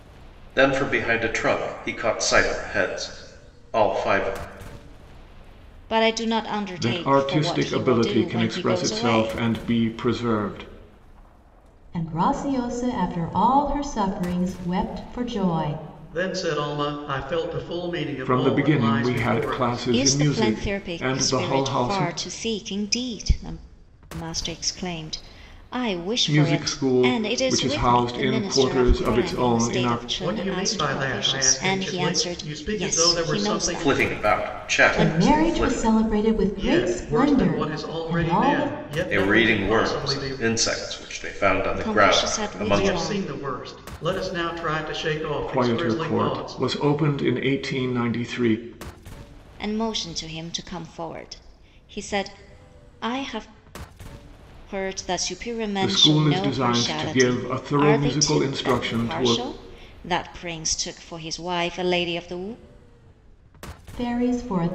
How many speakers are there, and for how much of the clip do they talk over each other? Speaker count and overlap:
five, about 40%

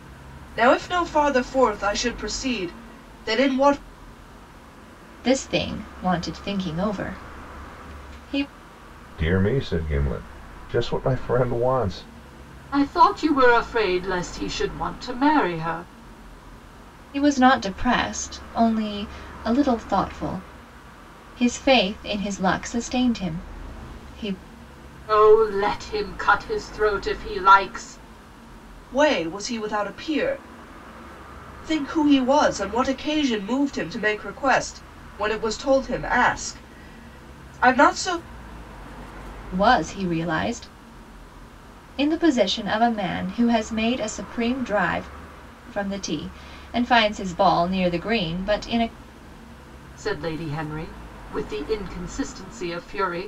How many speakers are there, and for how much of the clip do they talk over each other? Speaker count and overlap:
four, no overlap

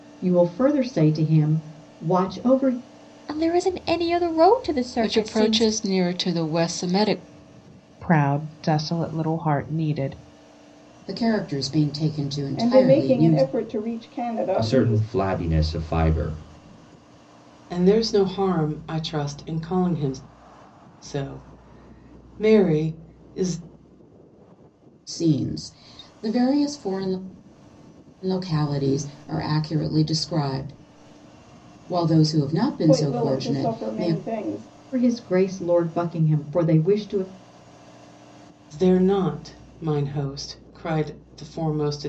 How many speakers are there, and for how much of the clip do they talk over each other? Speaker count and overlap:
eight, about 9%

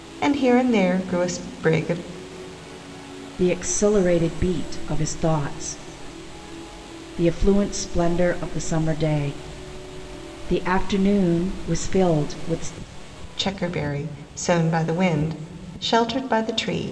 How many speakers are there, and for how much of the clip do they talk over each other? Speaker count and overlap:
two, no overlap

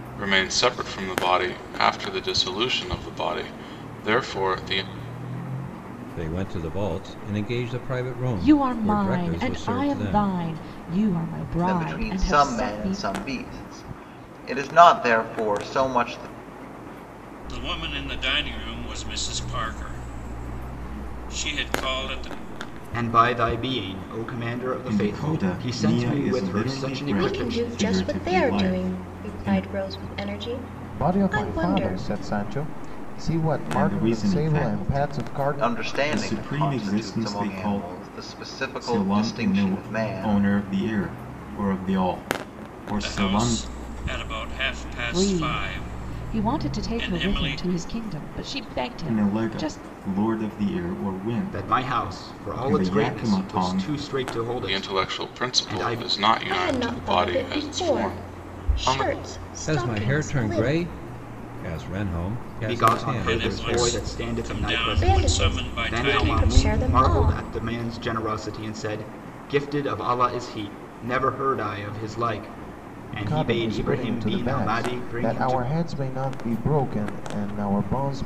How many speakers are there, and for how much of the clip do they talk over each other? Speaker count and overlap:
nine, about 44%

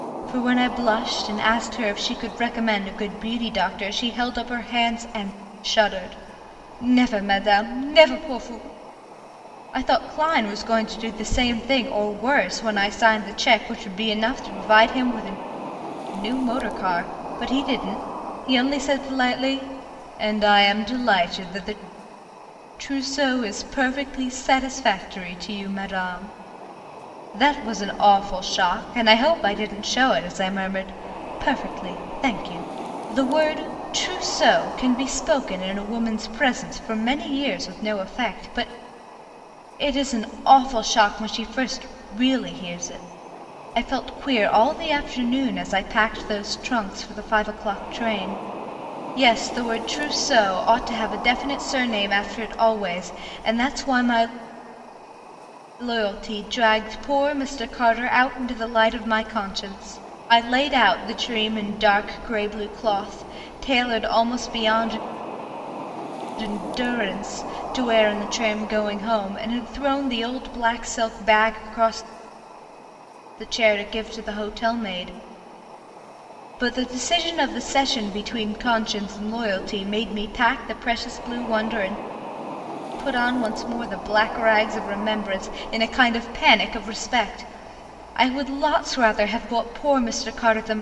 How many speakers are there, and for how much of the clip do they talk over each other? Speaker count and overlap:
one, no overlap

